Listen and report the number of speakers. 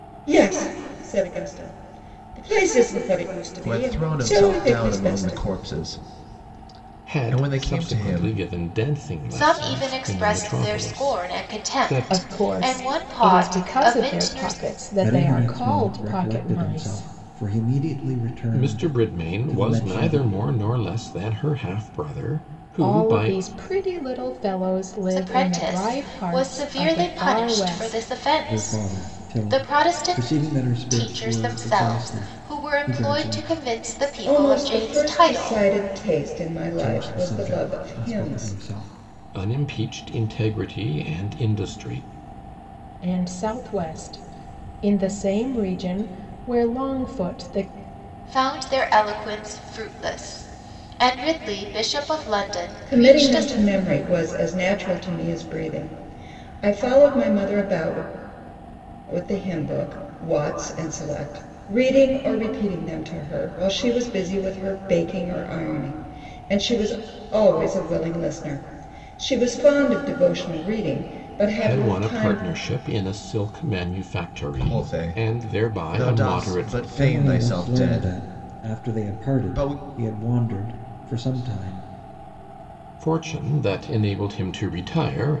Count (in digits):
6